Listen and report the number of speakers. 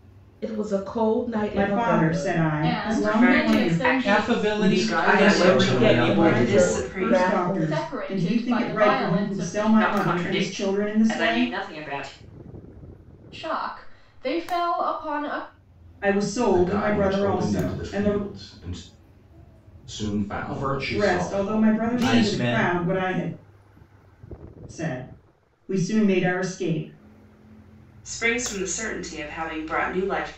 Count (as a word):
seven